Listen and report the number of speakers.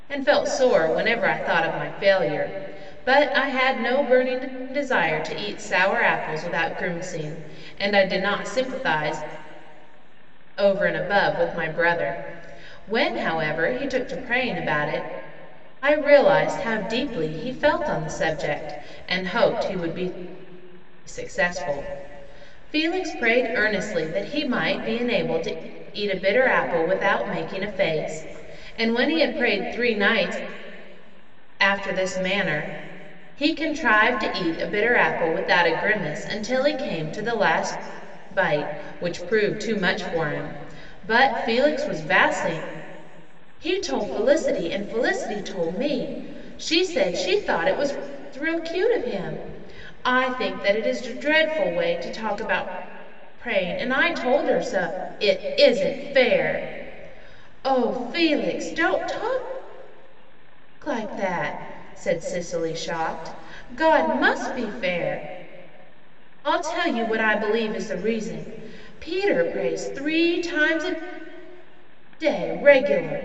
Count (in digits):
1